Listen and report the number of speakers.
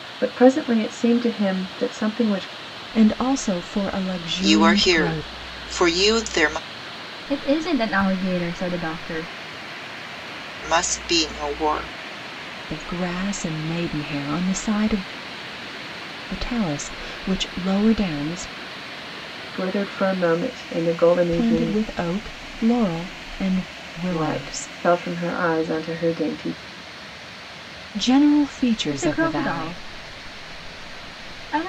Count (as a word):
four